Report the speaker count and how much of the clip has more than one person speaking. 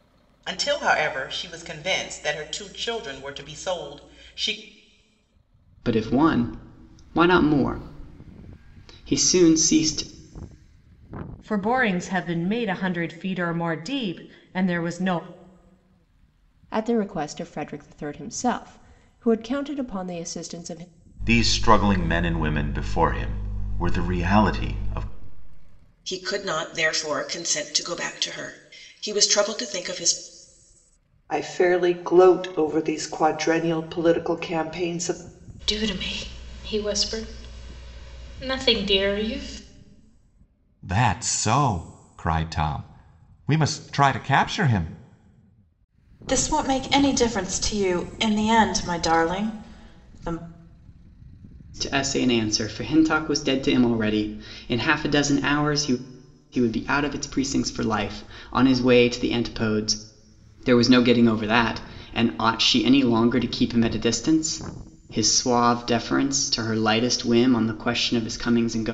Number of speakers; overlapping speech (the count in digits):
10, no overlap